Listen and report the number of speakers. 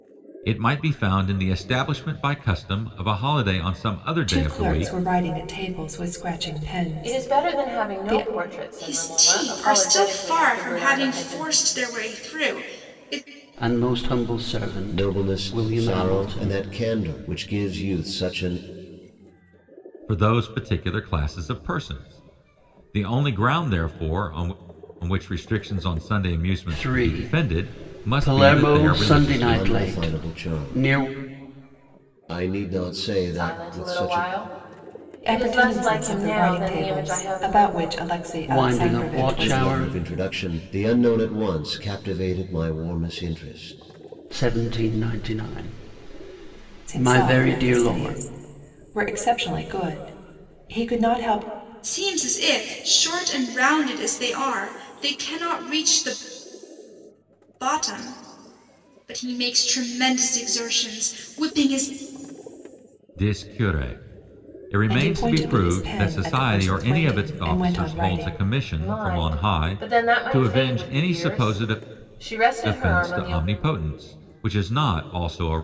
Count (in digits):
6